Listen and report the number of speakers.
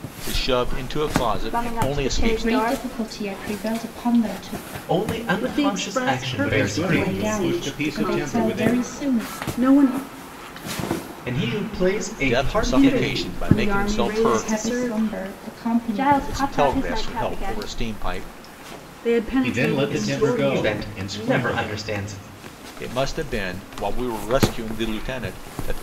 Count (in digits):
6